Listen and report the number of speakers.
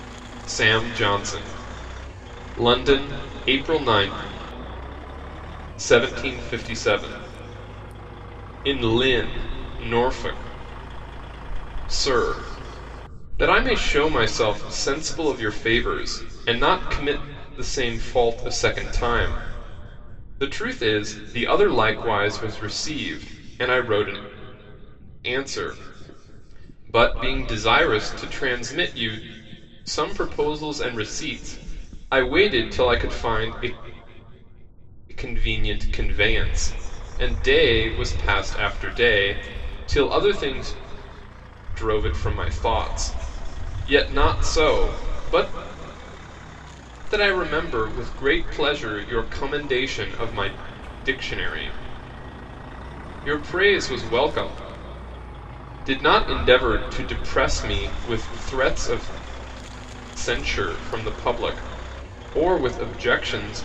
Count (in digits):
1